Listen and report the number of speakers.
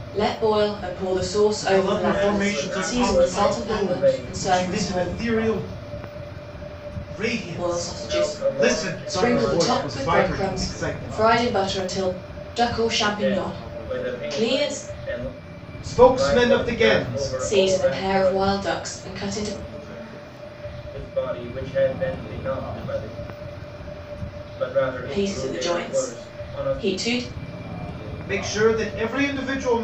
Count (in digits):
3